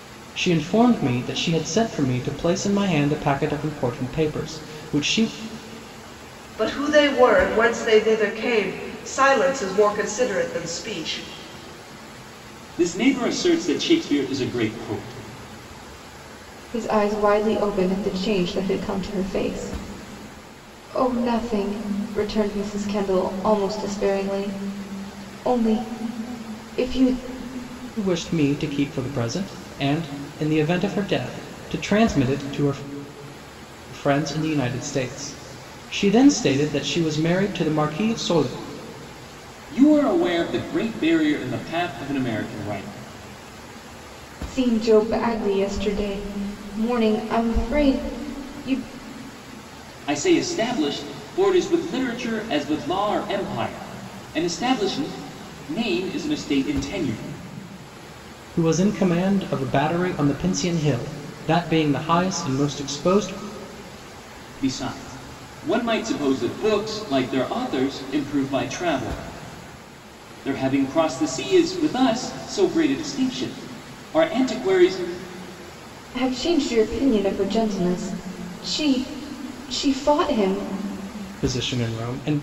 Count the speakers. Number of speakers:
four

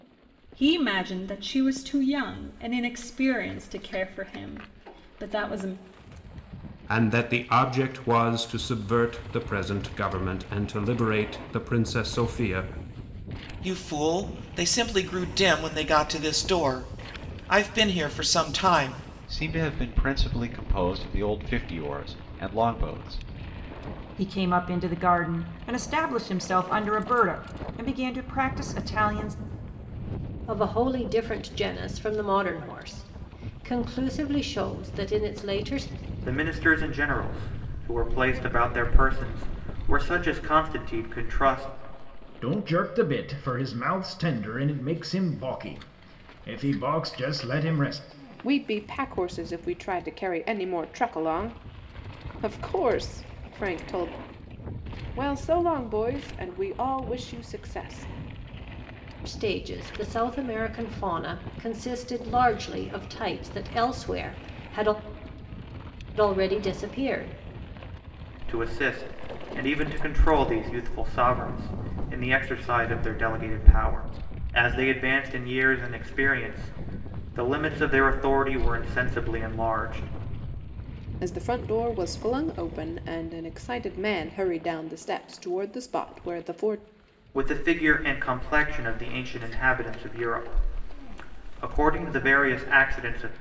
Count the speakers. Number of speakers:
nine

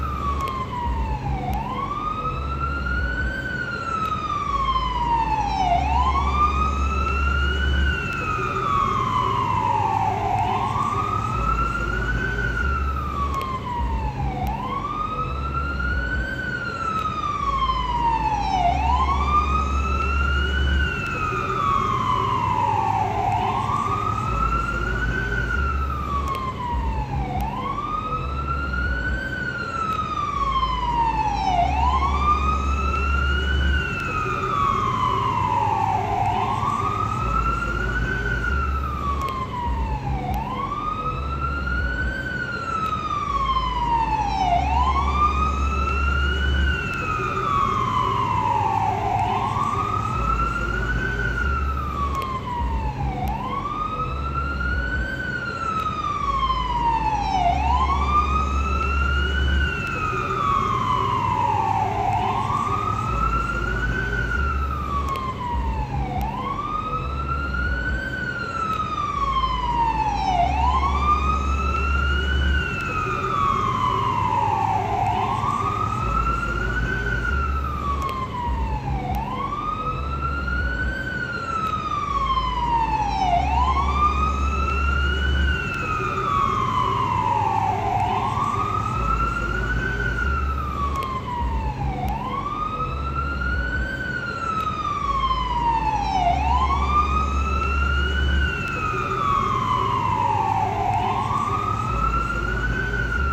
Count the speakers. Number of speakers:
zero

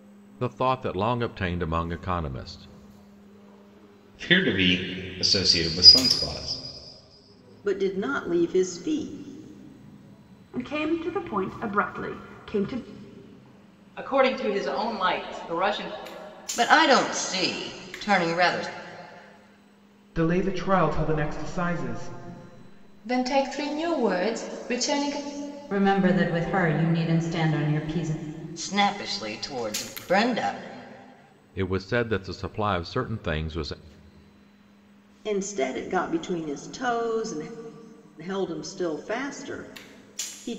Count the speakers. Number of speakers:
nine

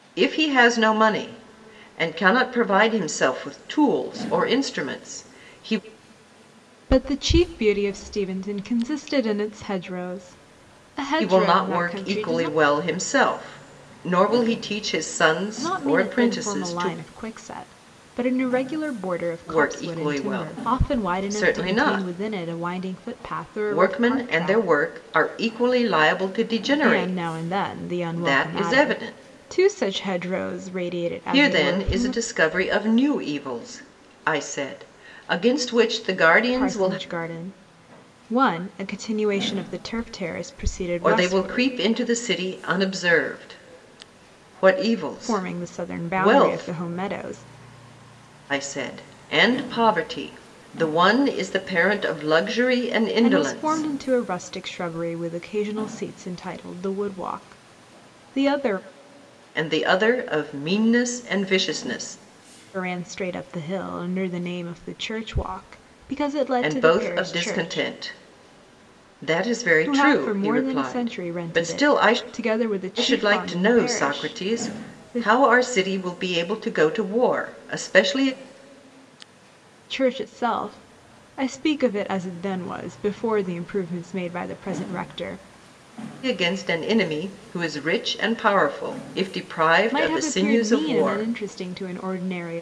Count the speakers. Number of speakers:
two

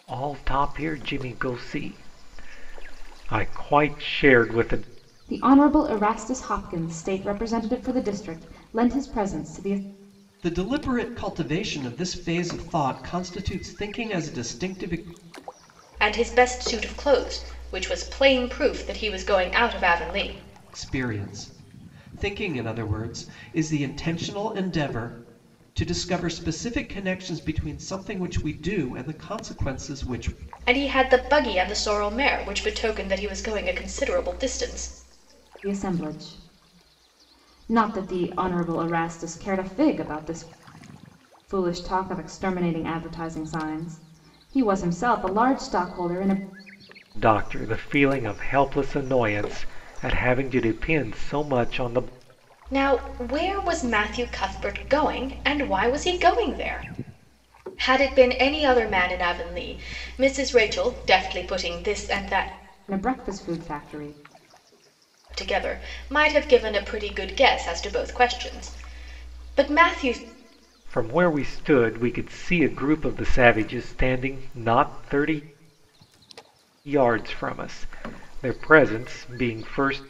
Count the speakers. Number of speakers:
four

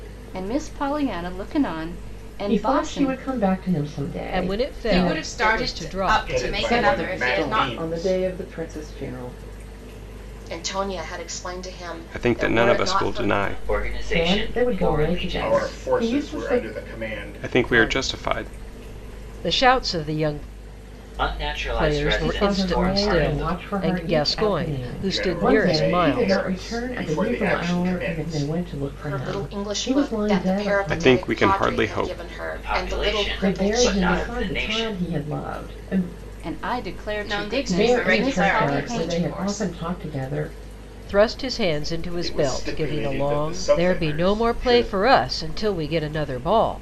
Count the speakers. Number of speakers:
ten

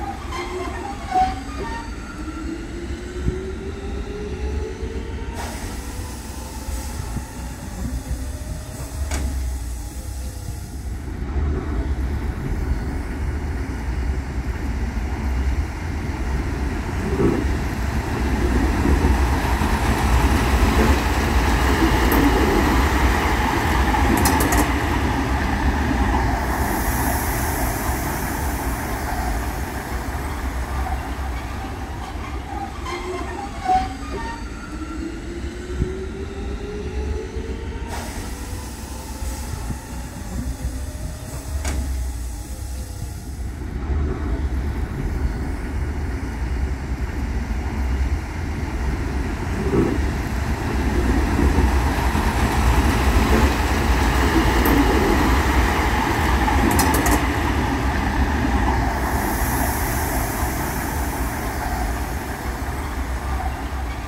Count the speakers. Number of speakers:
zero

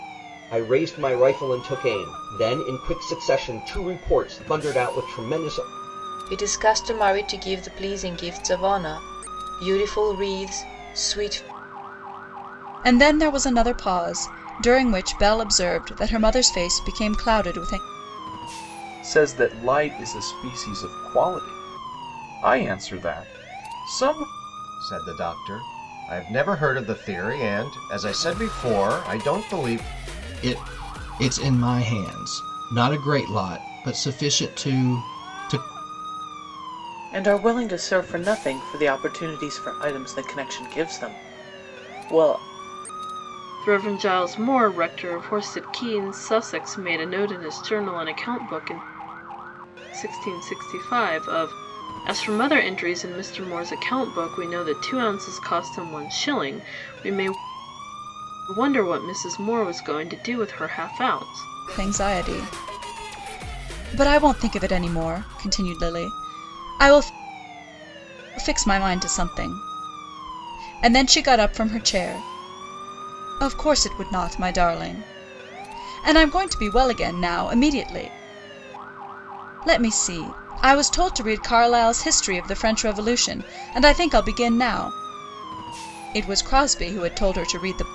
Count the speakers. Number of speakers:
eight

